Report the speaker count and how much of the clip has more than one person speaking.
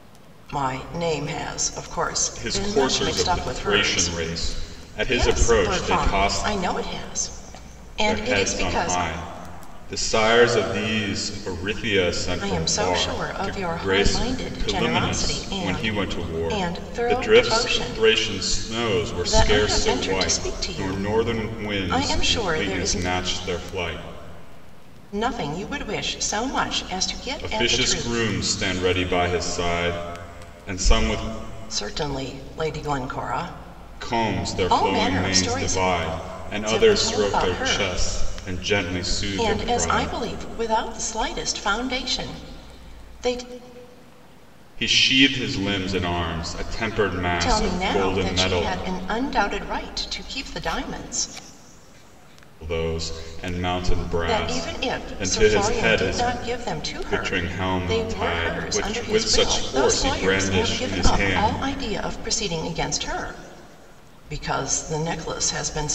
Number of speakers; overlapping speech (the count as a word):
two, about 39%